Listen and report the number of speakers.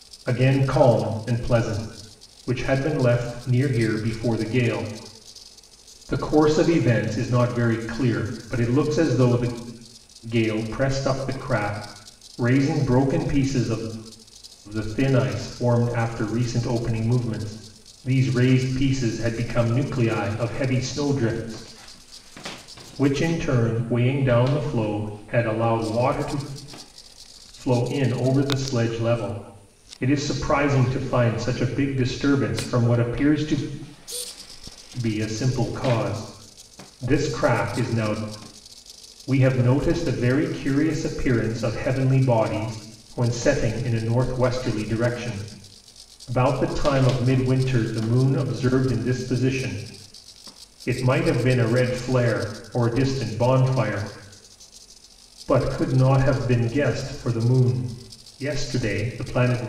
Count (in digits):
1